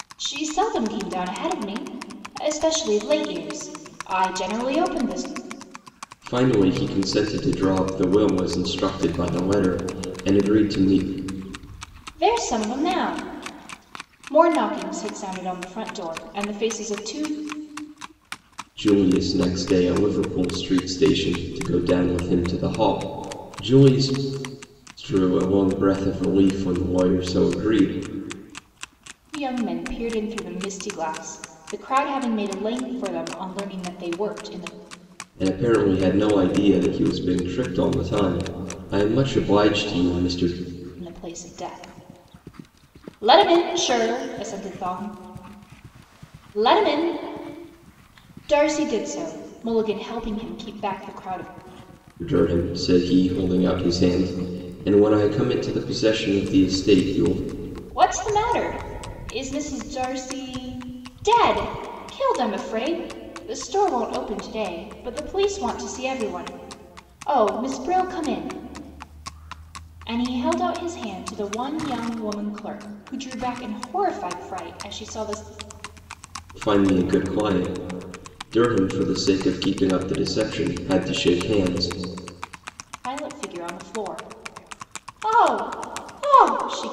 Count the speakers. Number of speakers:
2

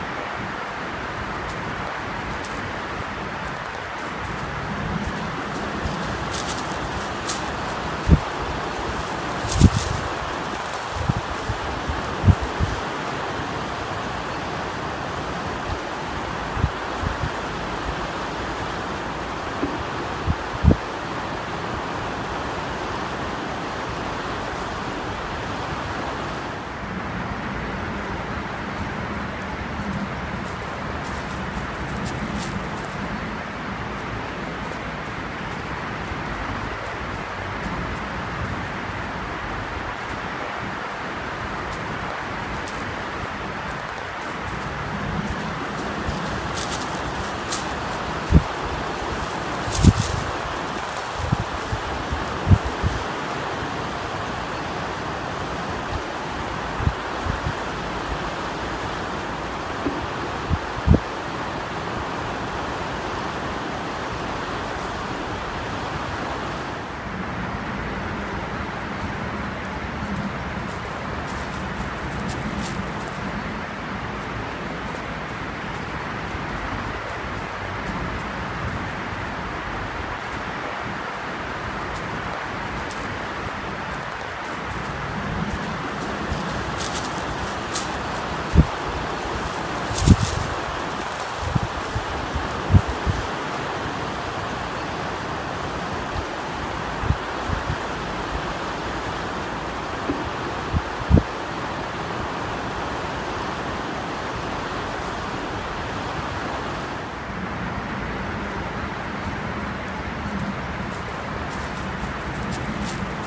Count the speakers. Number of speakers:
0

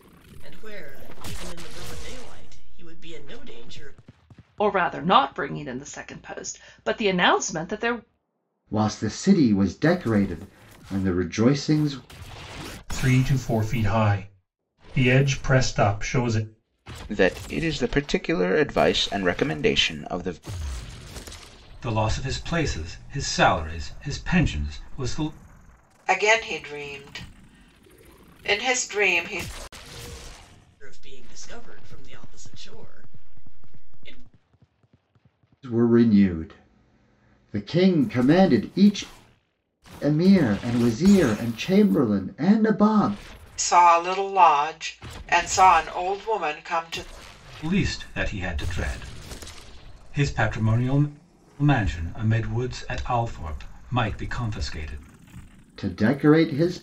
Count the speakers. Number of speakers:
7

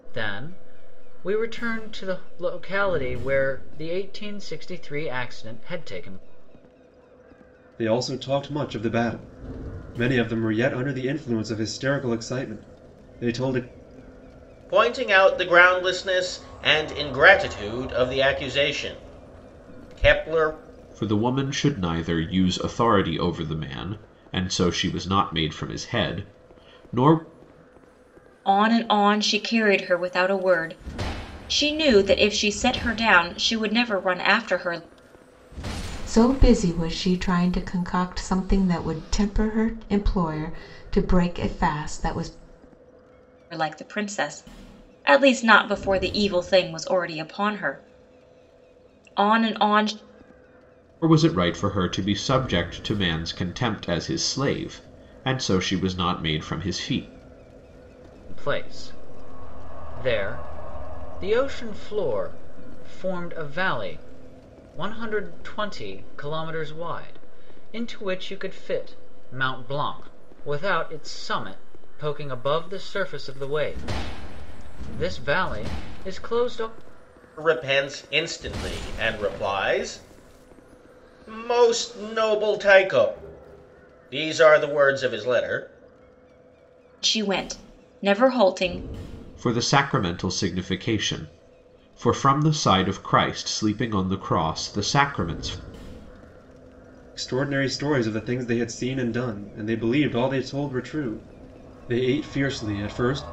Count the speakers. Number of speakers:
6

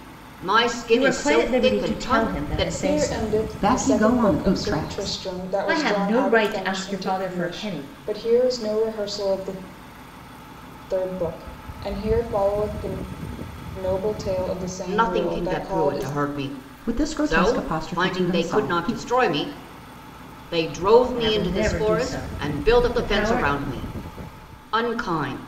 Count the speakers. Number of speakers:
4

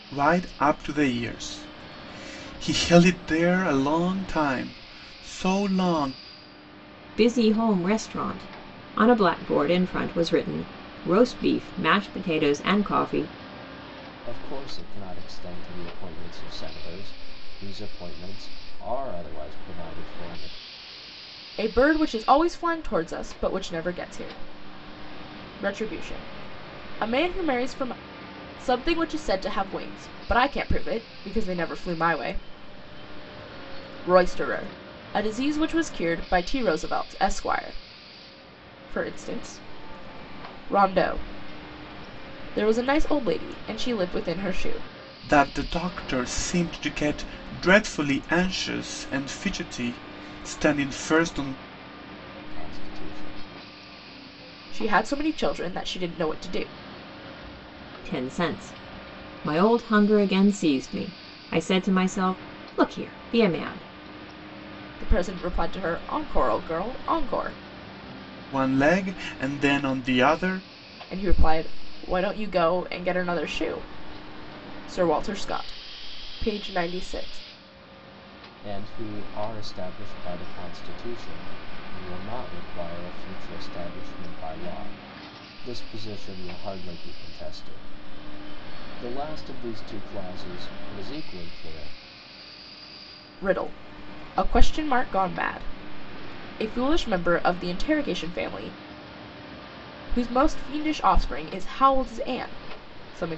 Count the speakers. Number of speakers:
4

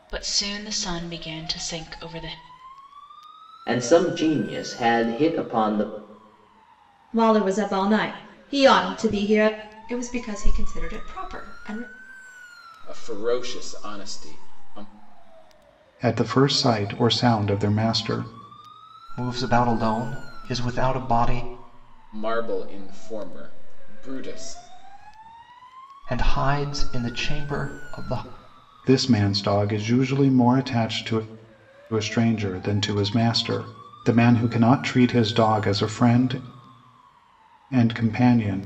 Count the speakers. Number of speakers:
7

